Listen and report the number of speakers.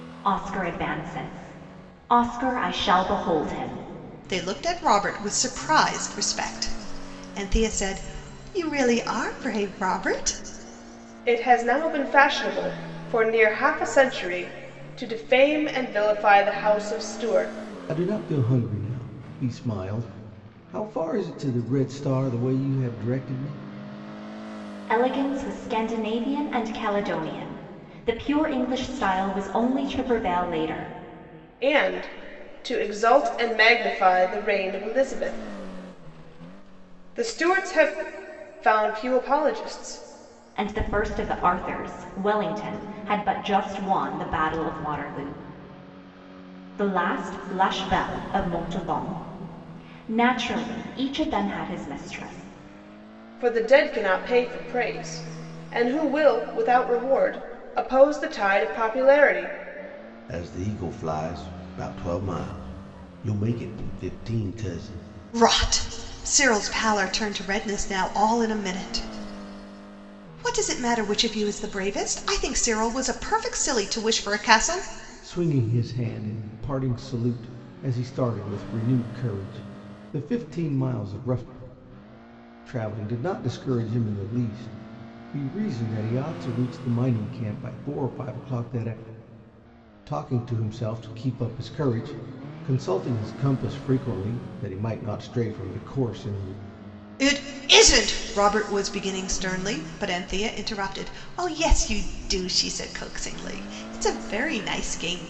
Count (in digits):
4